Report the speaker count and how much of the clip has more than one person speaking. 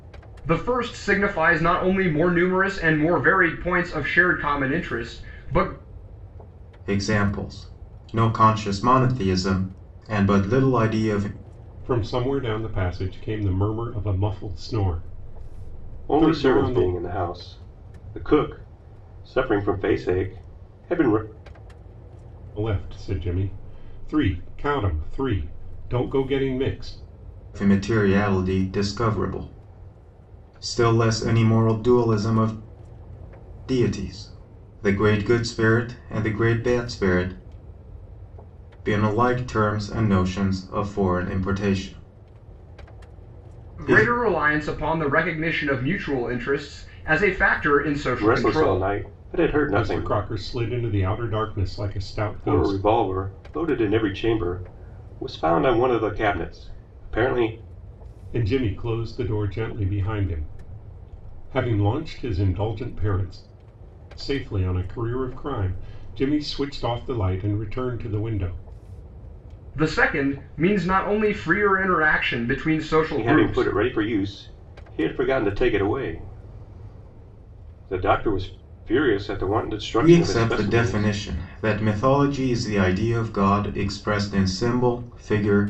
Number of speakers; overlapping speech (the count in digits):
4, about 5%